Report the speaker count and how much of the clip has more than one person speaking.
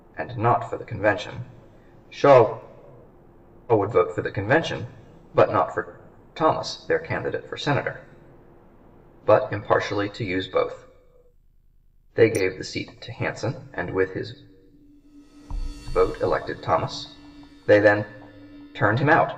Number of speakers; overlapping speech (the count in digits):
1, no overlap